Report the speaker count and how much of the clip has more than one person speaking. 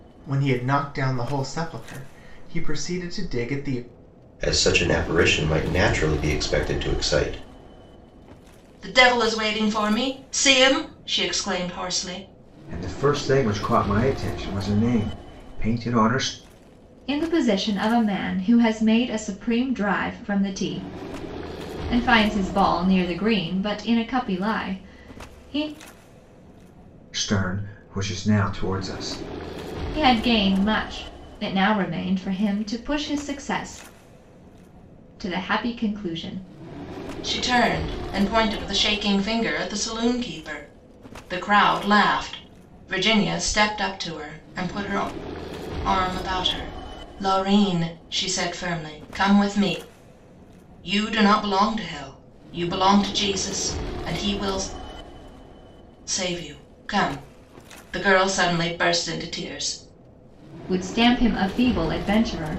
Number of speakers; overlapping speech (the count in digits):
5, no overlap